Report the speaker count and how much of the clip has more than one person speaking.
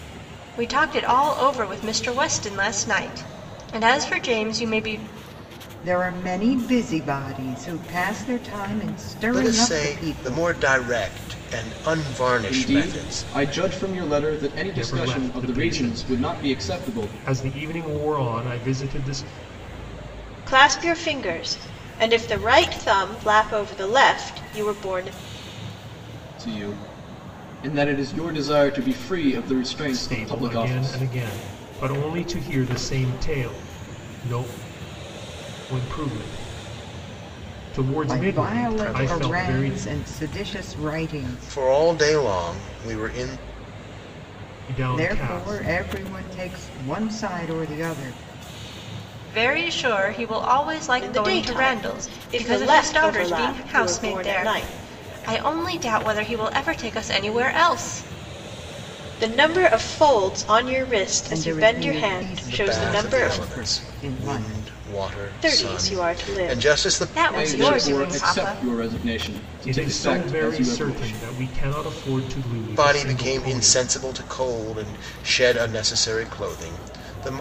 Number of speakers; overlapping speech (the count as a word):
six, about 30%